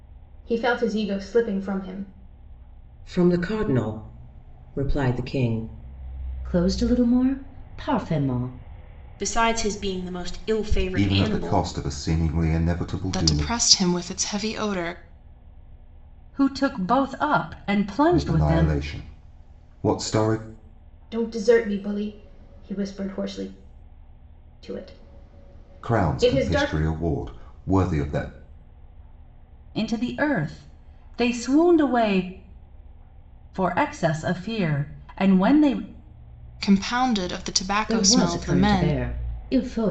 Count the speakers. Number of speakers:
seven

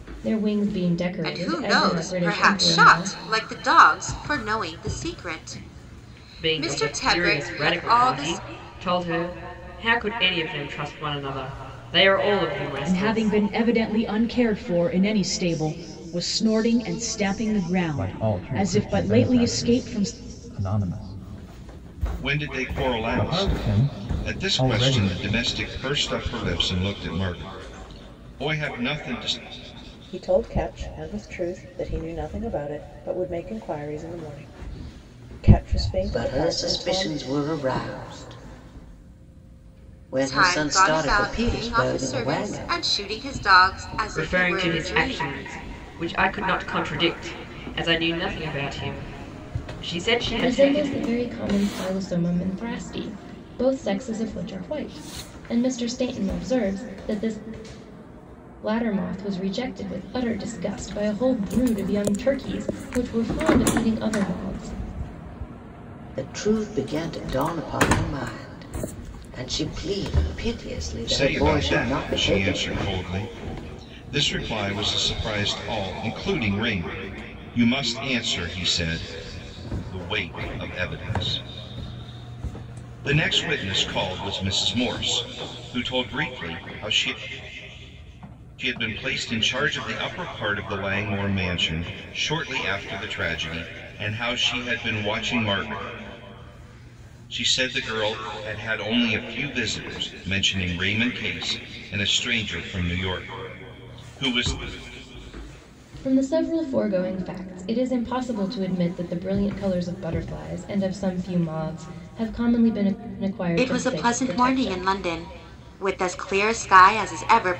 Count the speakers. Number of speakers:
eight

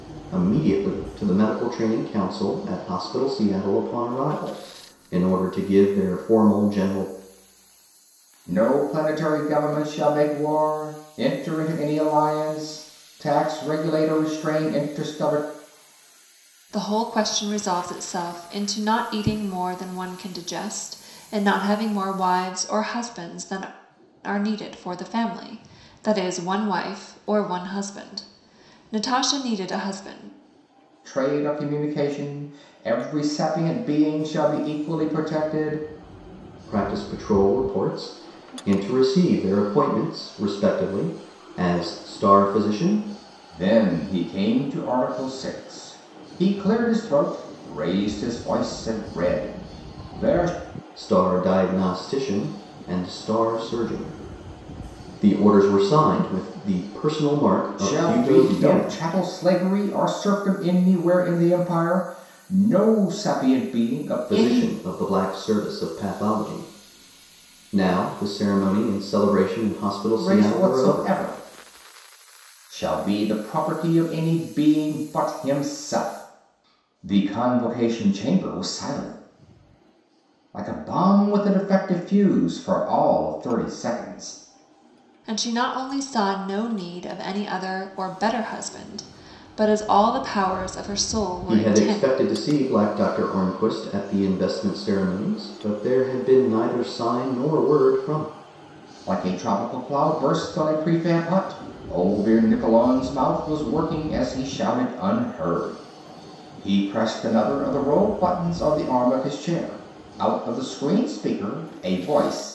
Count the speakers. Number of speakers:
three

